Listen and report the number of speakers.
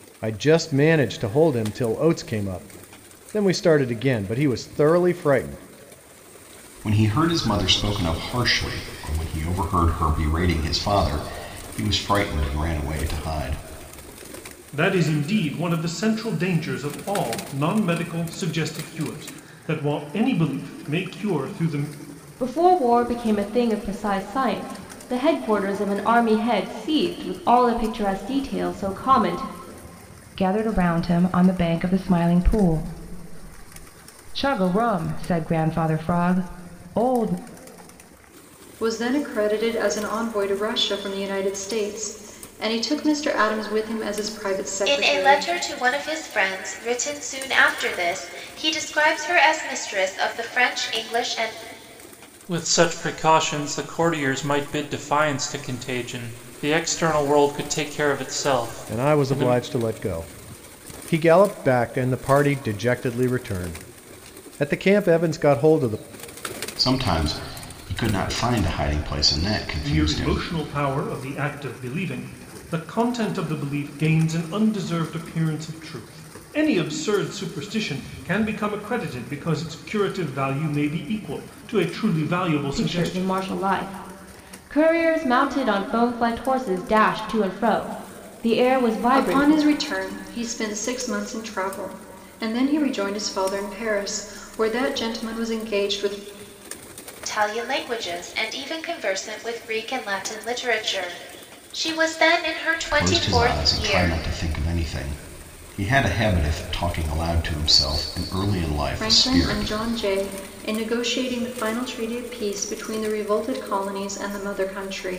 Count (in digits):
8